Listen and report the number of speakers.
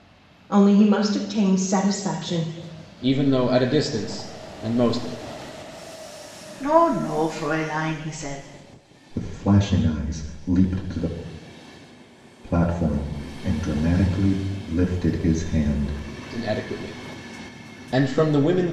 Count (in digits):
4